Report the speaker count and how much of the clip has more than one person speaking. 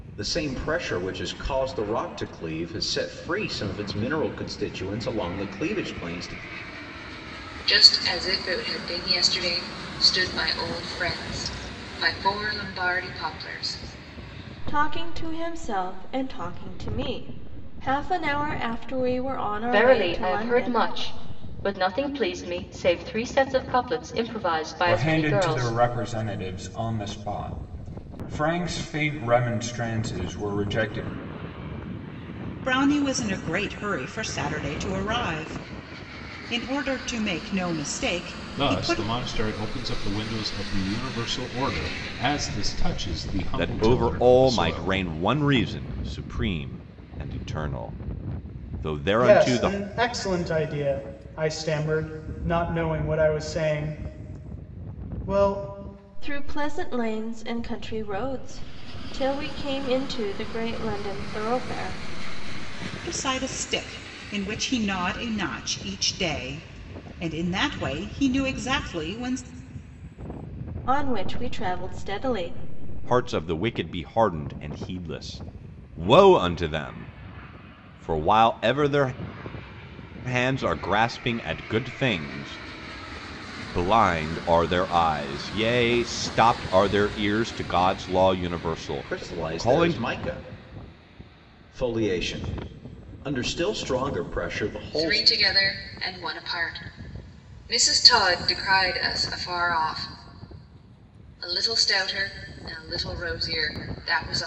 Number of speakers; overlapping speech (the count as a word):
nine, about 6%